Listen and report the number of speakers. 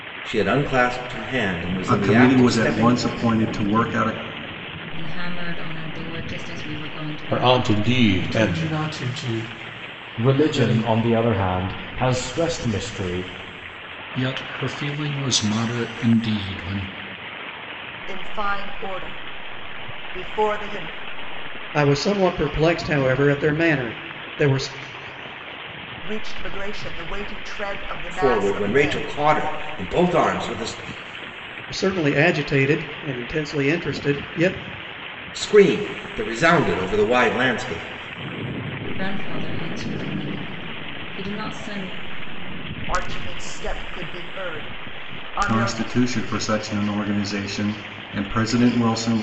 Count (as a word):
nine